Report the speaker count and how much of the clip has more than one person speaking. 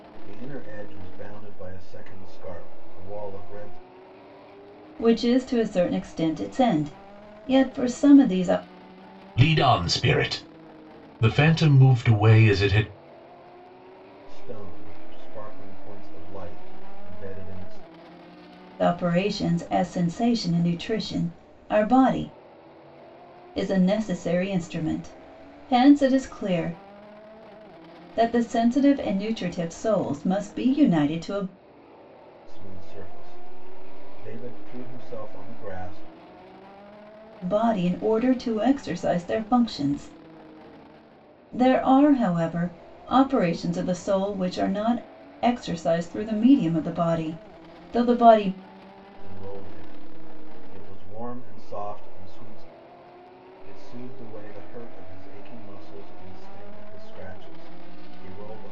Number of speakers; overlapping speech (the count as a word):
three, no overlap